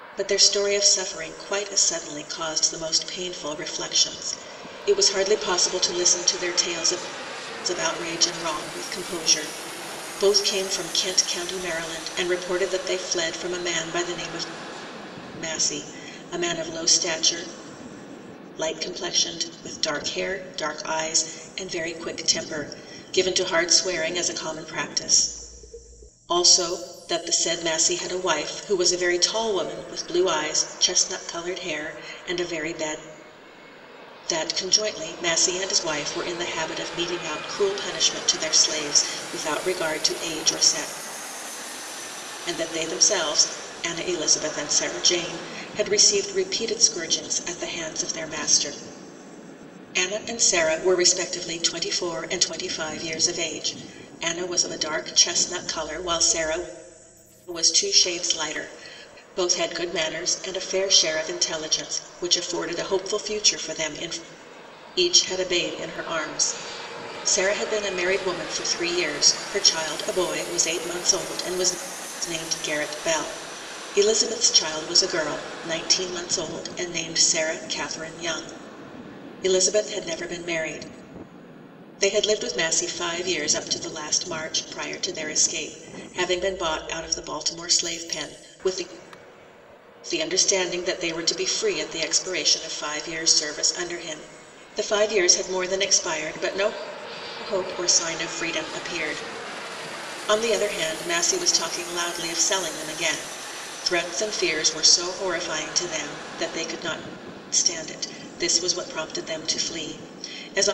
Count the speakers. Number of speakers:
one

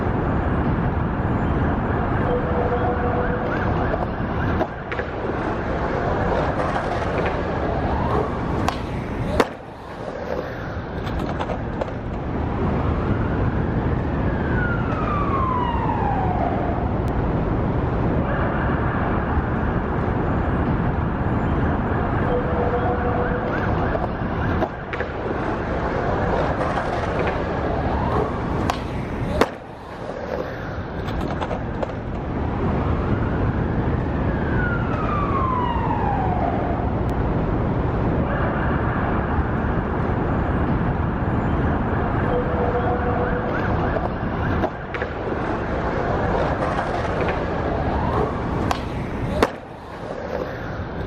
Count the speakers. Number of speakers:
zero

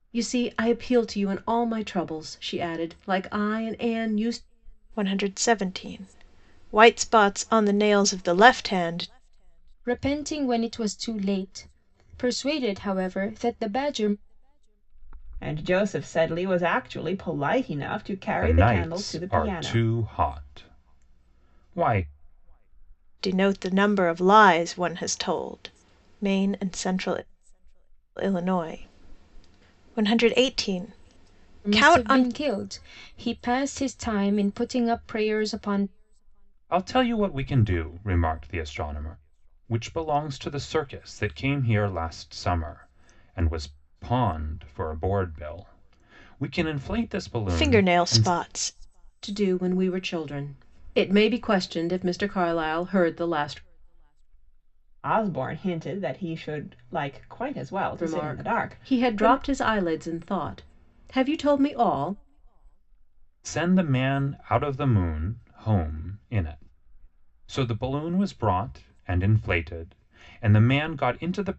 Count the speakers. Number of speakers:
five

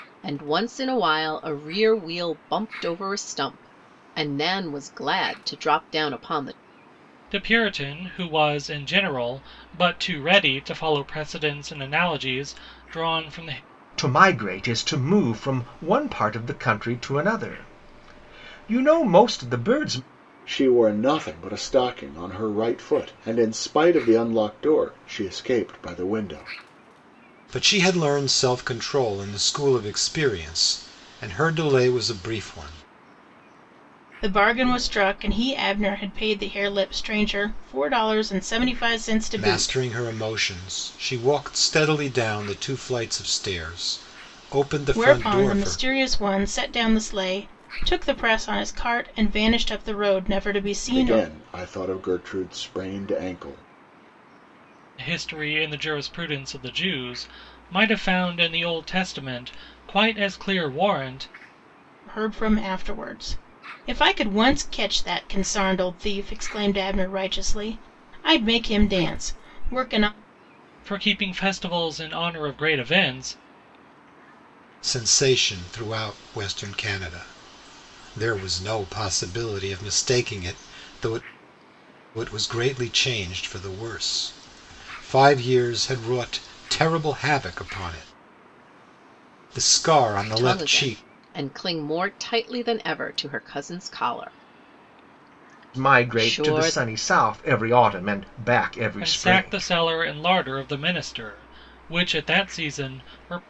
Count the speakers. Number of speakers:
six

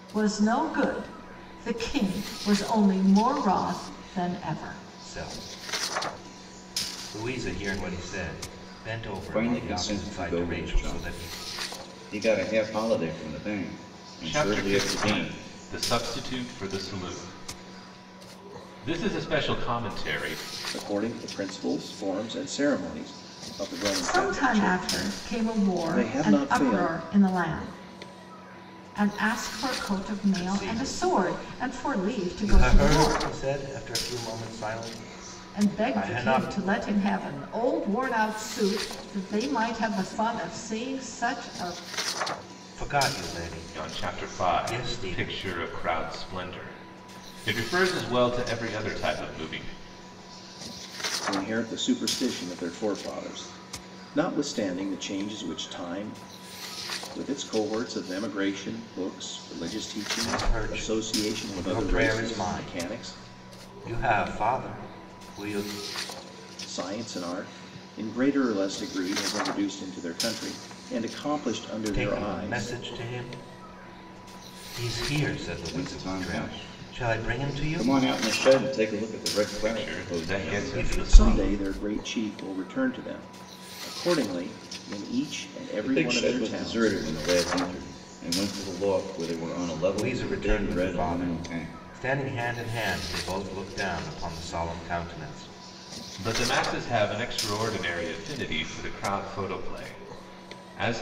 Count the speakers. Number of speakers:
five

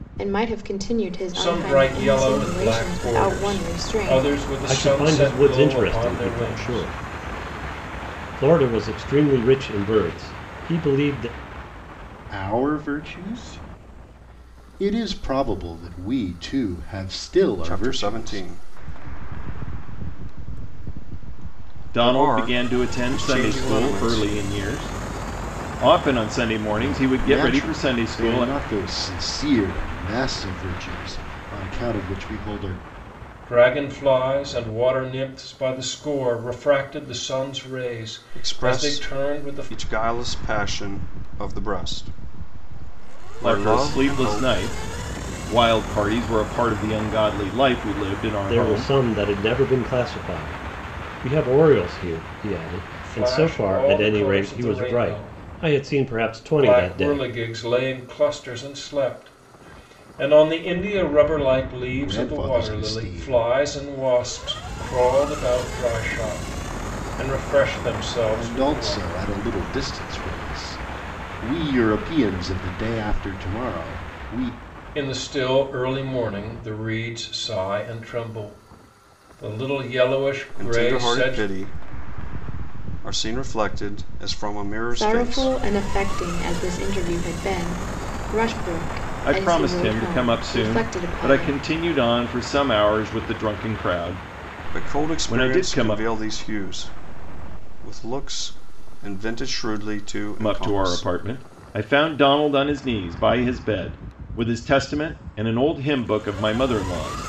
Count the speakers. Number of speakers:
six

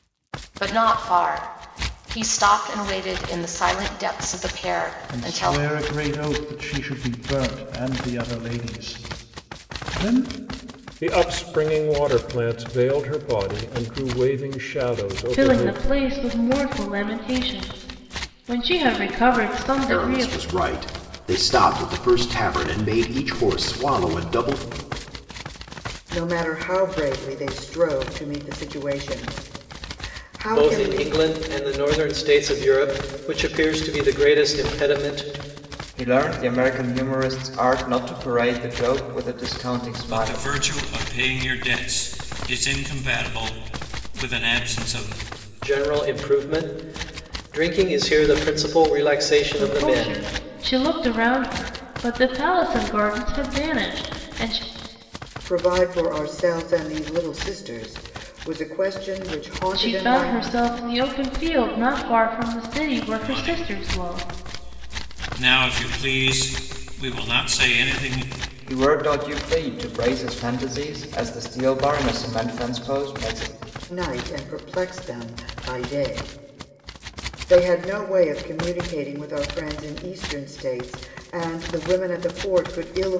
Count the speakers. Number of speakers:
nine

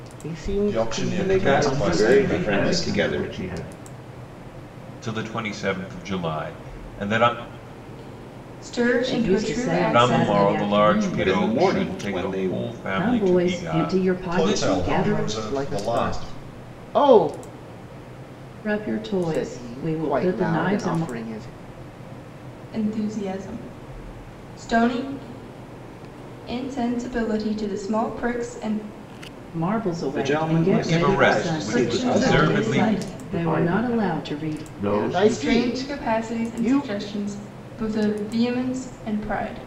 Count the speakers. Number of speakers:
seven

